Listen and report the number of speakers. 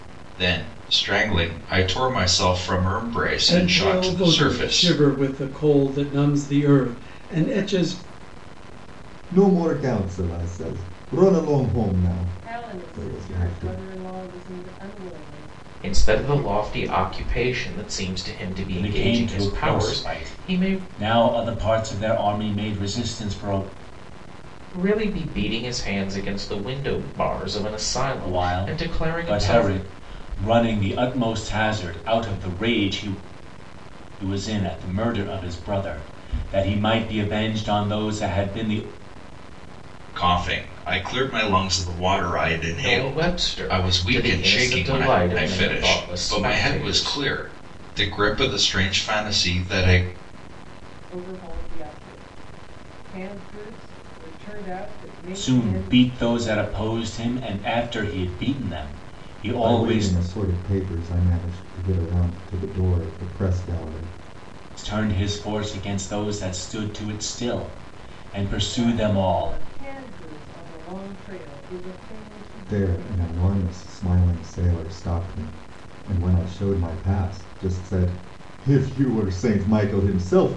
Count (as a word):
six